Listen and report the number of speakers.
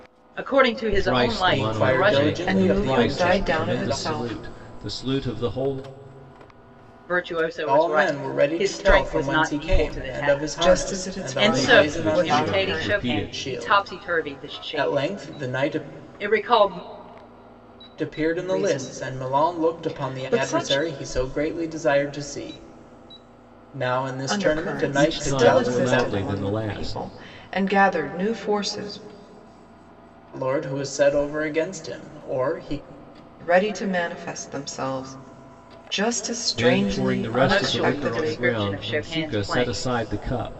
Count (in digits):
4